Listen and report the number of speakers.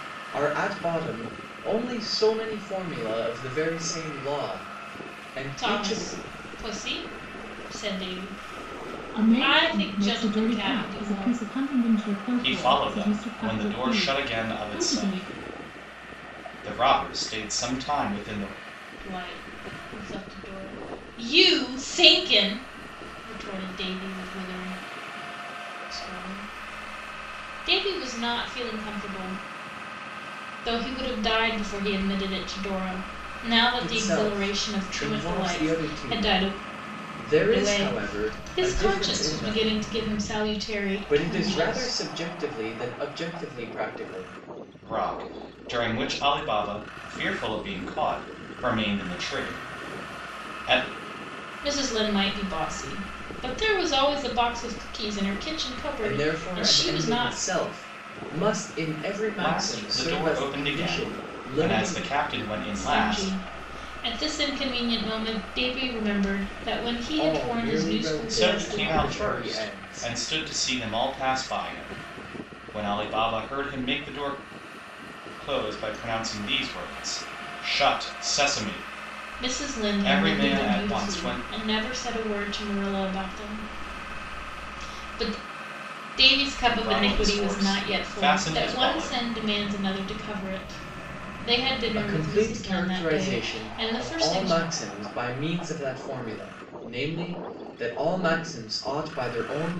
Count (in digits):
4